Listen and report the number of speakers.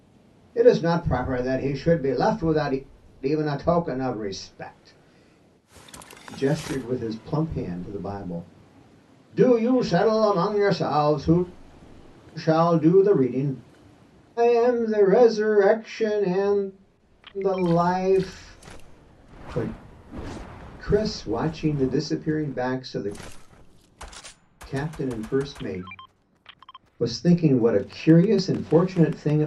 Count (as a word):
one